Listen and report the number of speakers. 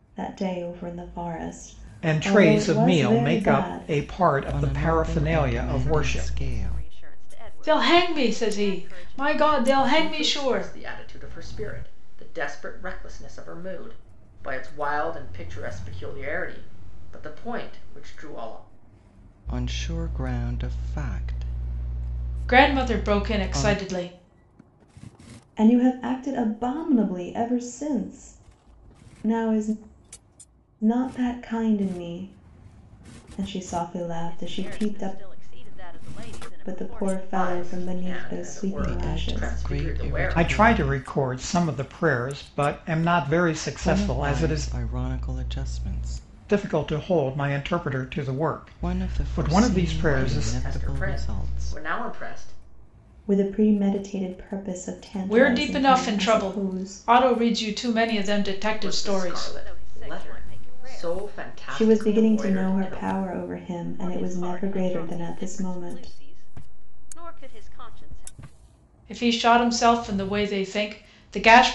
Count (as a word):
six